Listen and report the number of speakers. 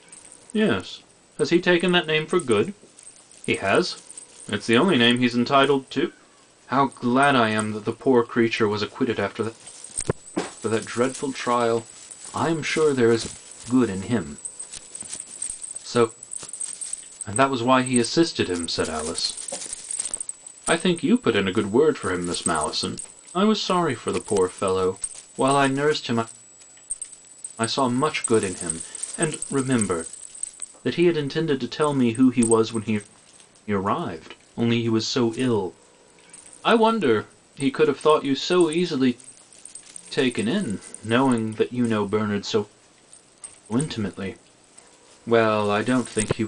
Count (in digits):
1